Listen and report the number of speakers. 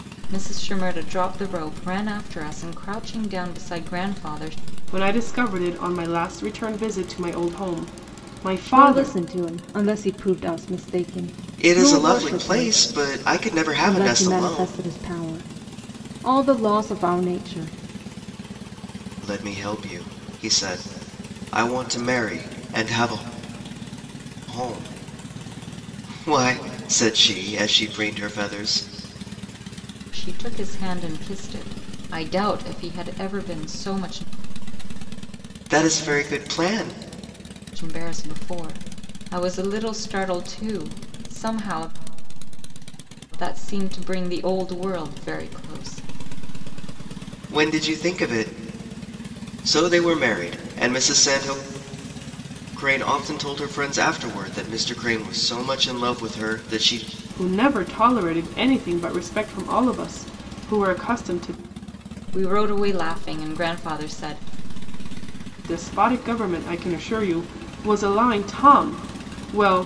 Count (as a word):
four